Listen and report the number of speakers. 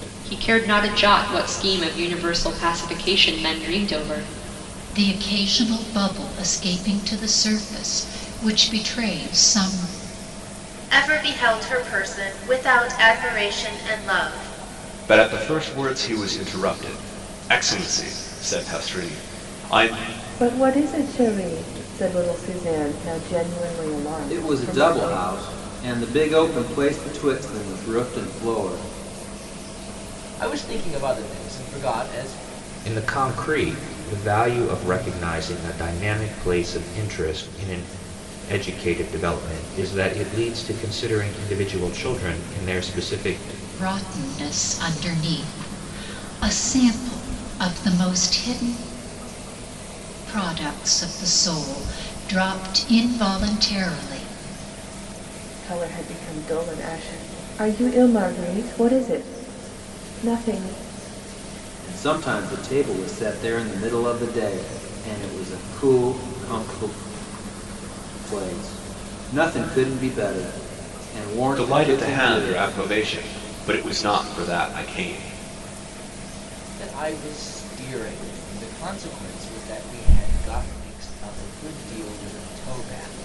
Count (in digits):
8